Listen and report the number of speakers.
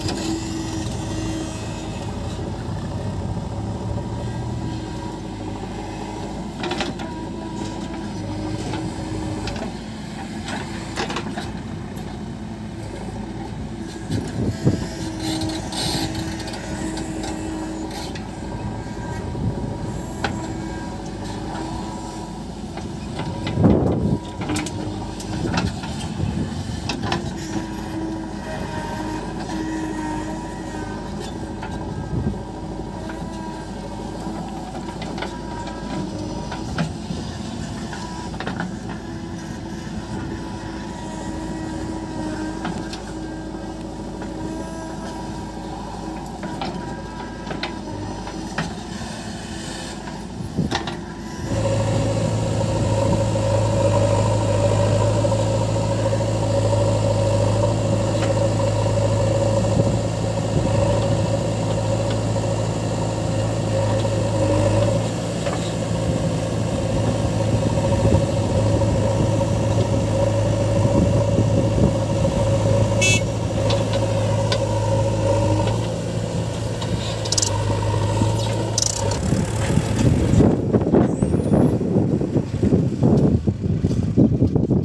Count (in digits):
0